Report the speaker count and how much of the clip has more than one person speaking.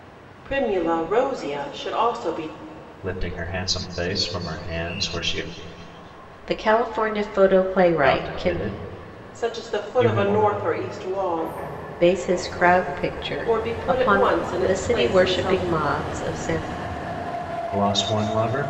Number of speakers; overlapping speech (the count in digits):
3, about 19%